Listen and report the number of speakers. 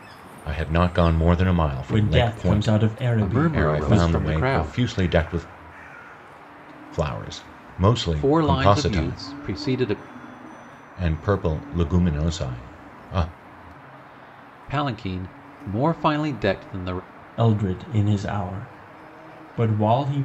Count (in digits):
3